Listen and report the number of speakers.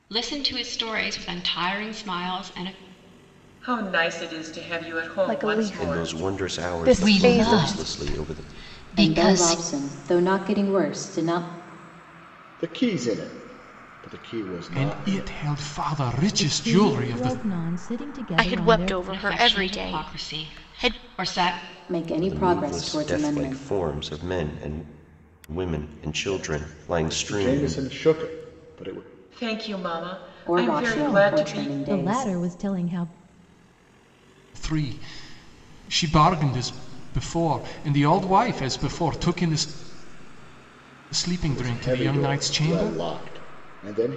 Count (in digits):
10